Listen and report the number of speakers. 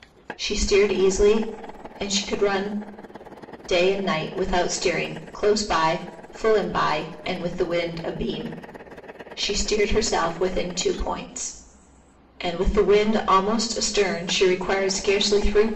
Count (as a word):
one